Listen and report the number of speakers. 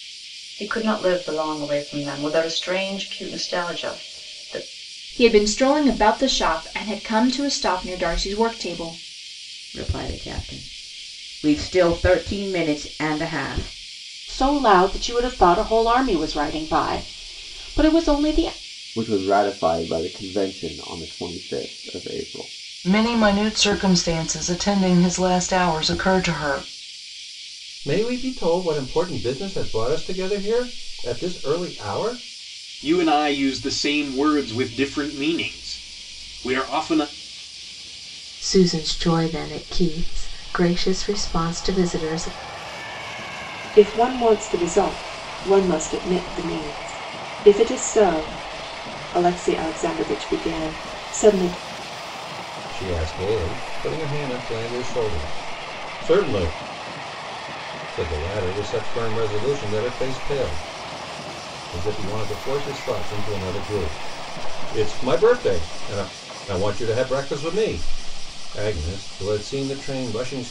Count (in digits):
10